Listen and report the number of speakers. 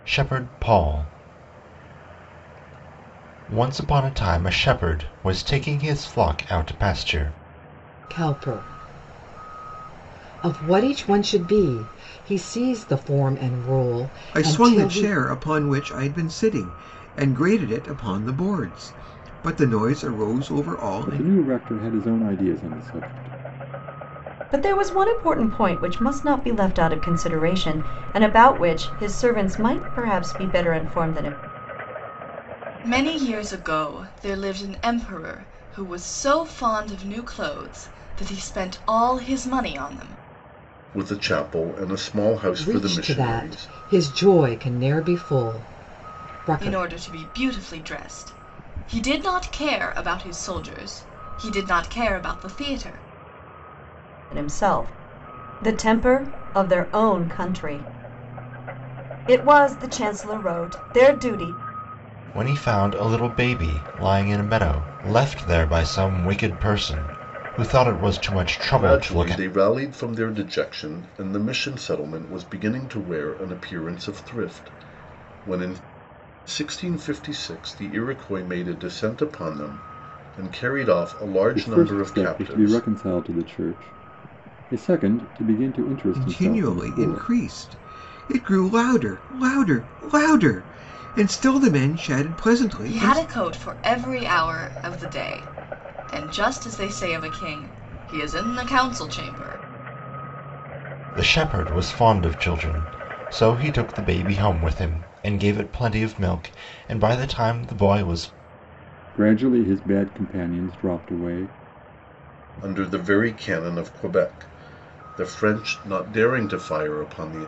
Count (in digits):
7